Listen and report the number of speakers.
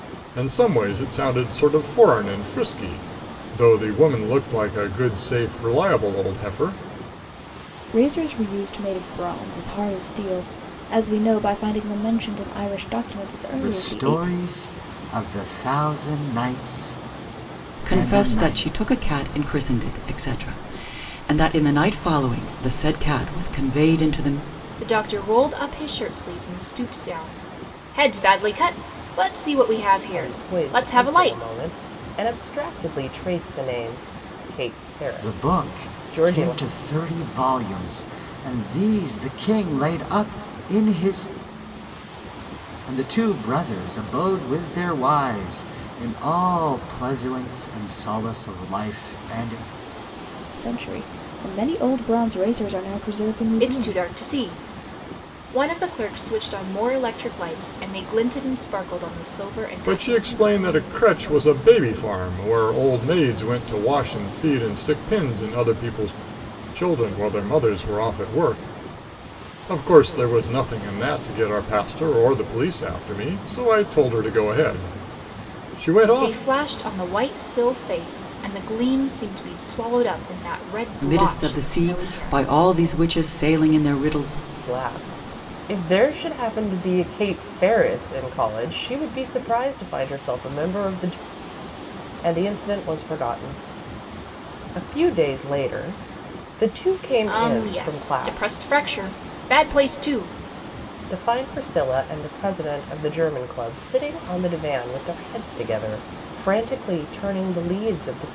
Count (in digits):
6